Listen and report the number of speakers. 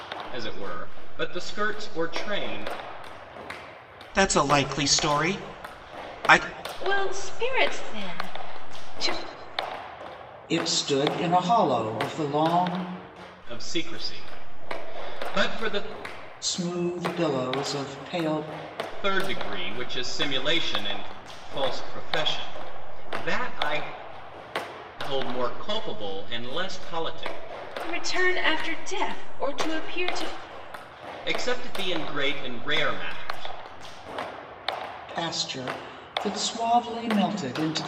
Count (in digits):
4